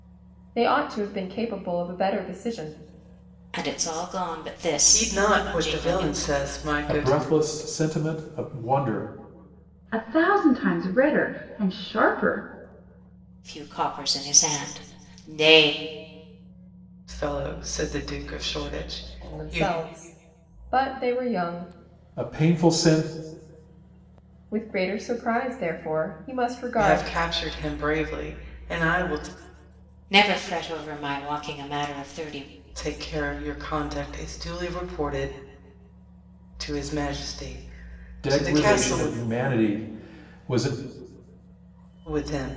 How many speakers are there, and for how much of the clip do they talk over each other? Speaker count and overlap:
5, about 8%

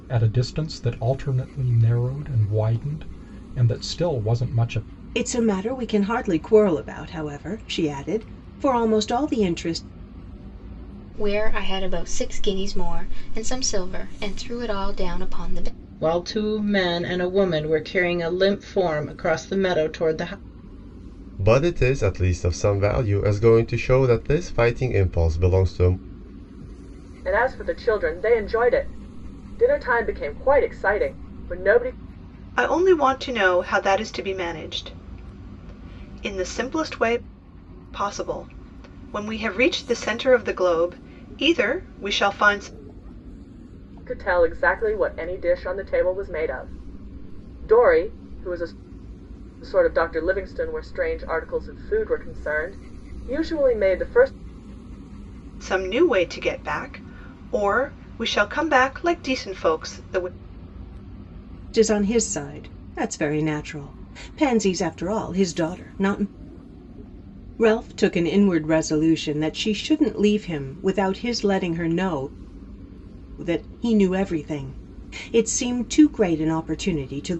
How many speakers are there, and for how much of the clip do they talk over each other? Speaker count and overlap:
7, no overlap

